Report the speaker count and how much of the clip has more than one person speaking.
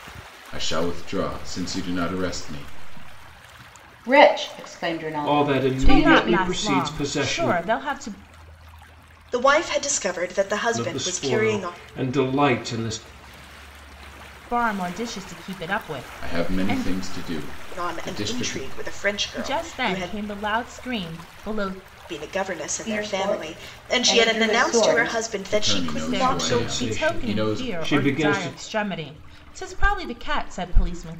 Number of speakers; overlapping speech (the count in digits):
5, about 36%